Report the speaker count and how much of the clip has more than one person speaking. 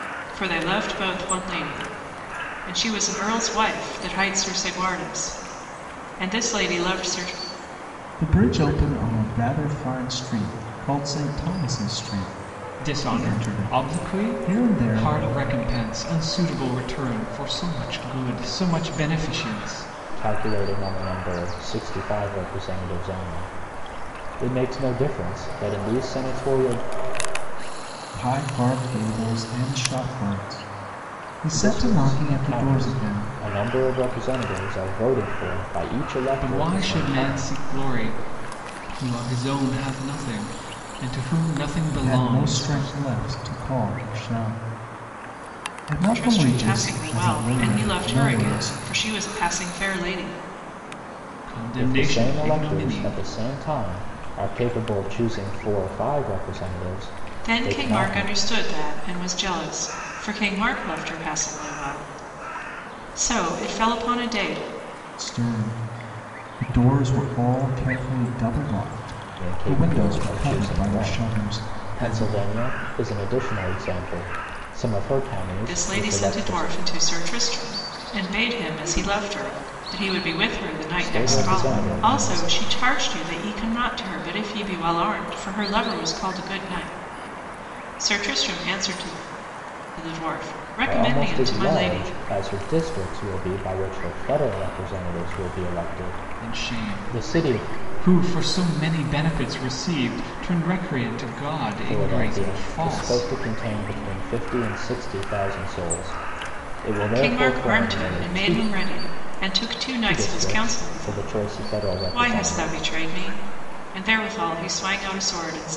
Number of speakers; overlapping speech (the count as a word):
four, about 21%